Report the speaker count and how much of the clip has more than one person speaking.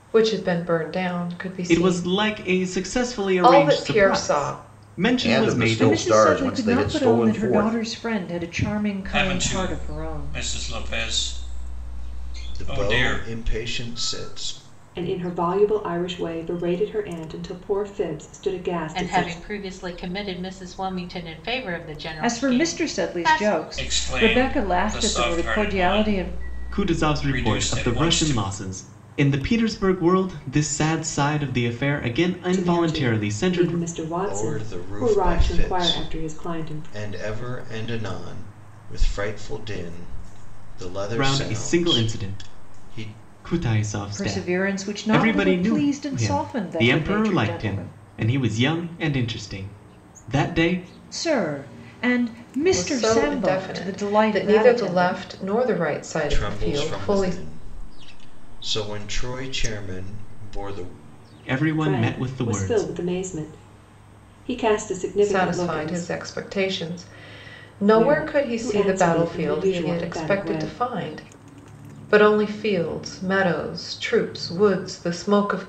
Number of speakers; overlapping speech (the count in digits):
8, about 43%